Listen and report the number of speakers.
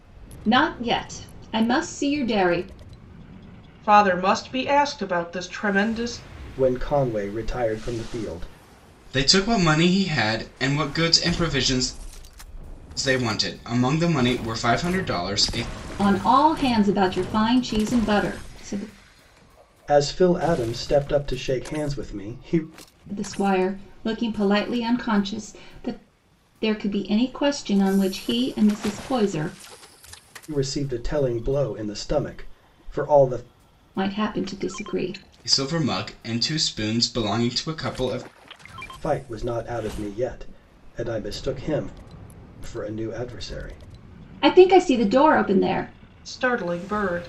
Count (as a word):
four